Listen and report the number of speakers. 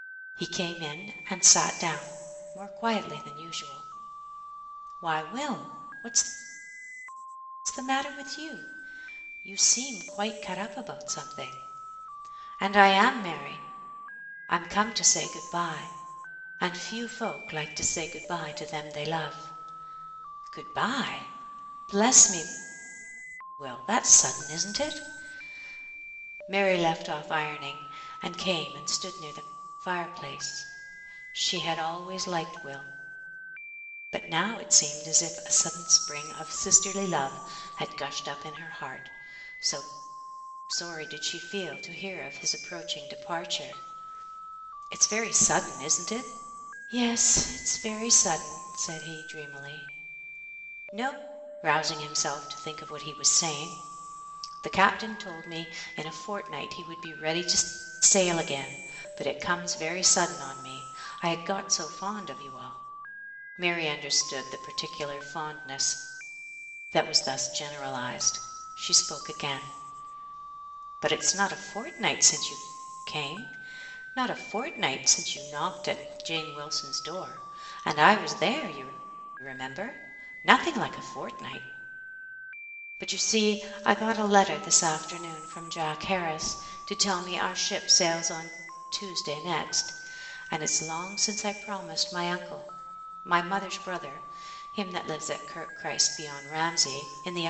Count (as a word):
one